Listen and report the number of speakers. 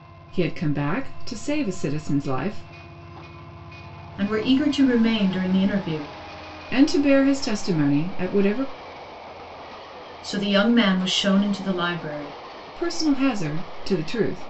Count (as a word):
two